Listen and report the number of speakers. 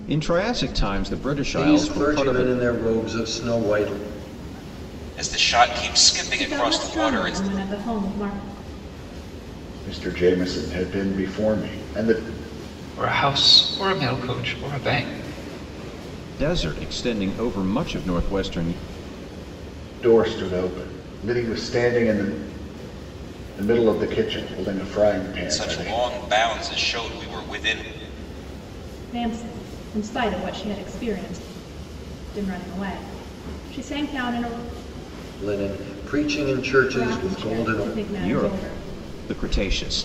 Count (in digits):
6